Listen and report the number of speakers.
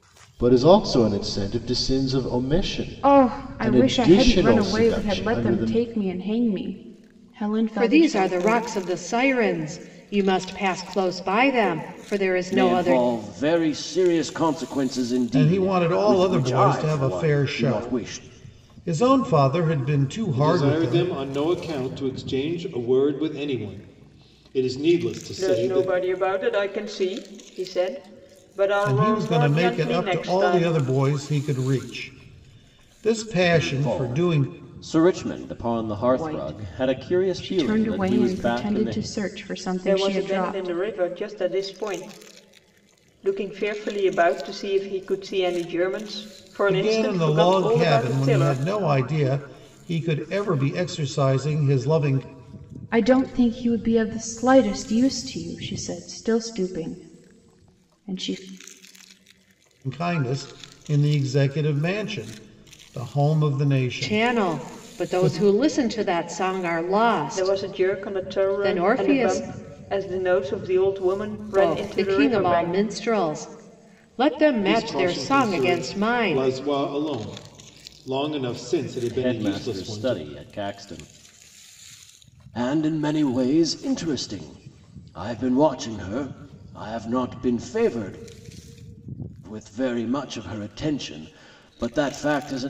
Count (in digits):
7